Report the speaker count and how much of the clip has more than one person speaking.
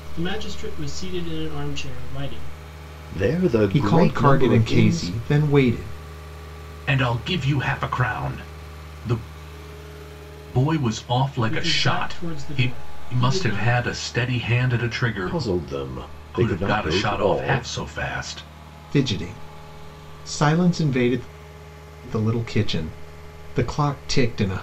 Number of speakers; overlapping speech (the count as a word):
four, about 21%